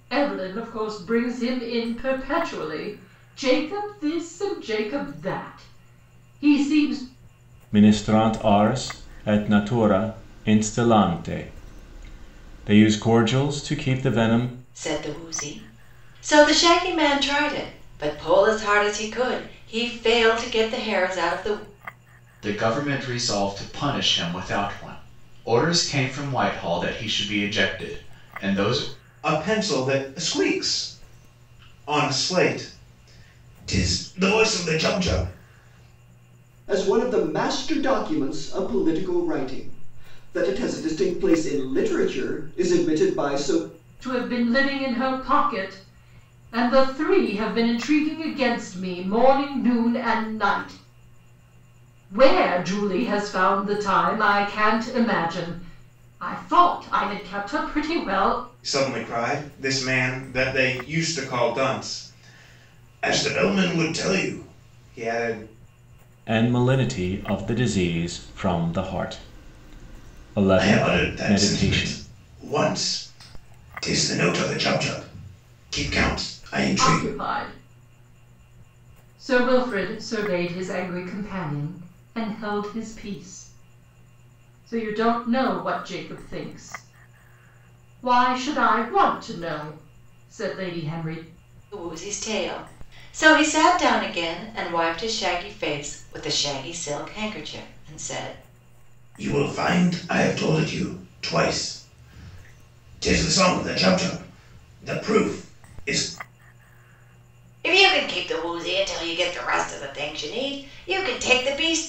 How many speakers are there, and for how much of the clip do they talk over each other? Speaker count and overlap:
six, about 2%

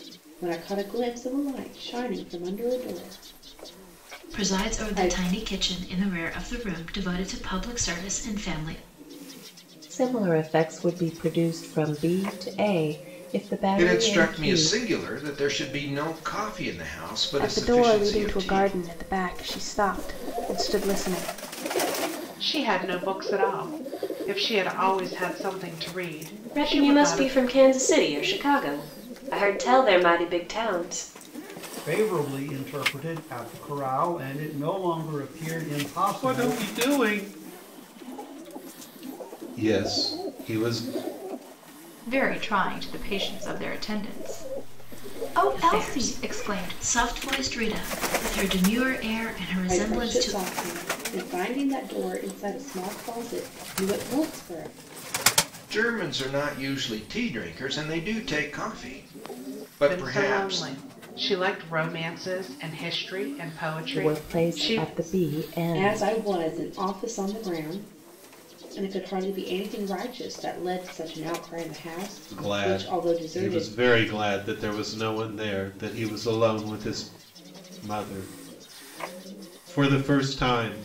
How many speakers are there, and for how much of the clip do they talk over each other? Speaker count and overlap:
ten, about 14%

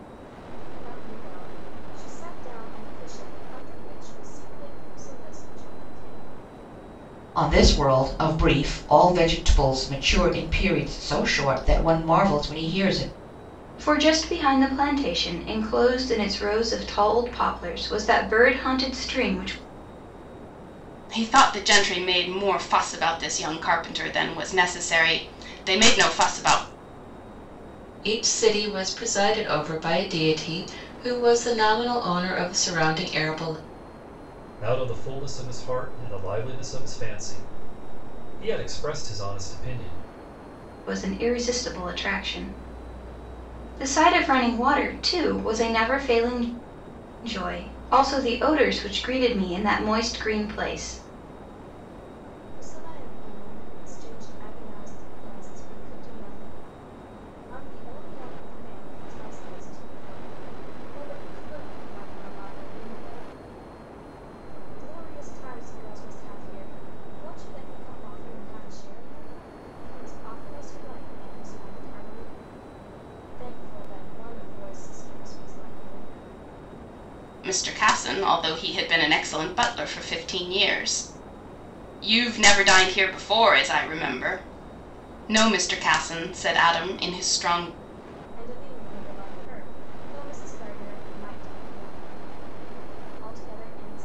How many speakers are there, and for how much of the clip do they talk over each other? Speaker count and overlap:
six, no overlap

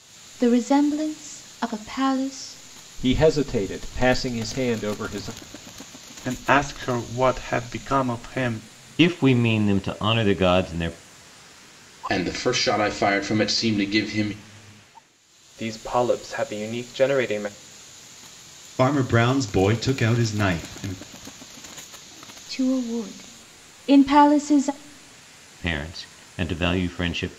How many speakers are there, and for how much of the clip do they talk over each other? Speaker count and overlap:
seven, no overlap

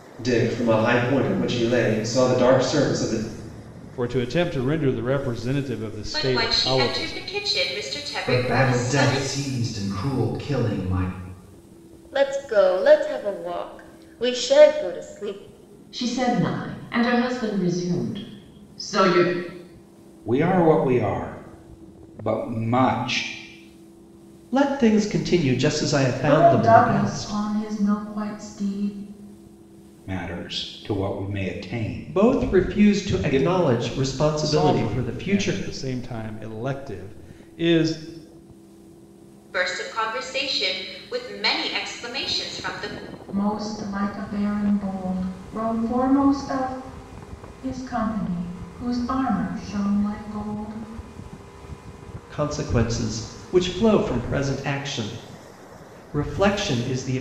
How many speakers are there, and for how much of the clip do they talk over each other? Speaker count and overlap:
nine, about 11%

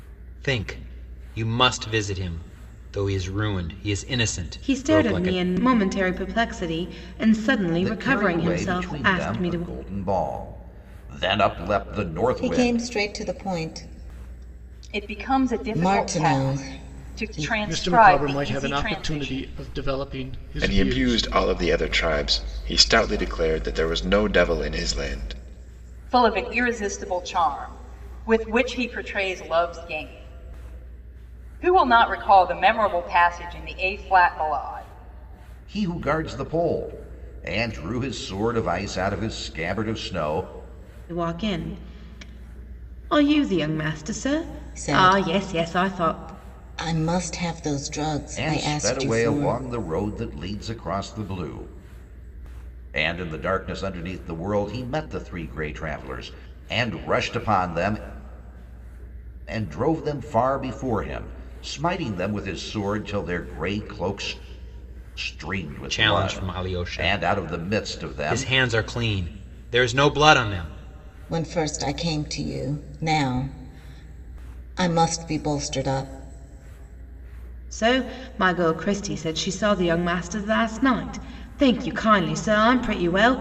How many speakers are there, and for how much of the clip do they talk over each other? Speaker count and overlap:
seven, about 17%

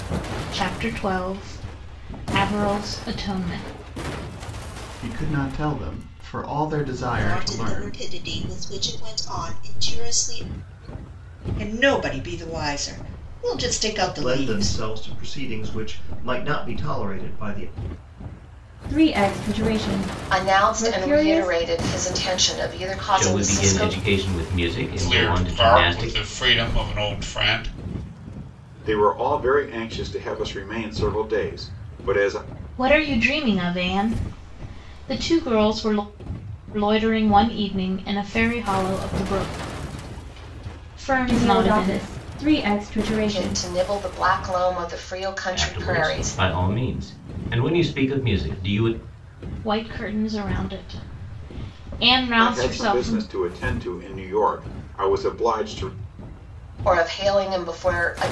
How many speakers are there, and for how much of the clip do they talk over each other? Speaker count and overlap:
ten, about 14%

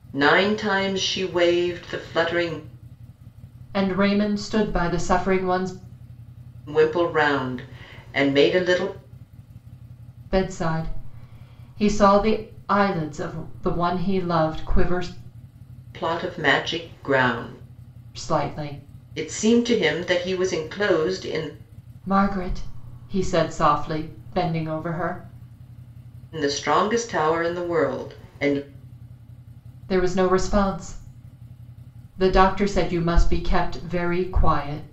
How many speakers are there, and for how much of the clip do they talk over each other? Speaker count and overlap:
two, no overlap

